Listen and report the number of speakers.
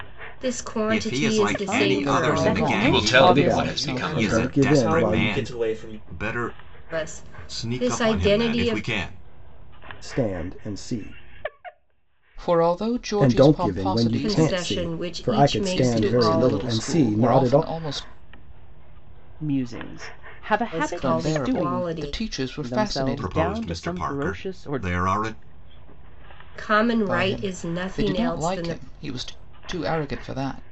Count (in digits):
7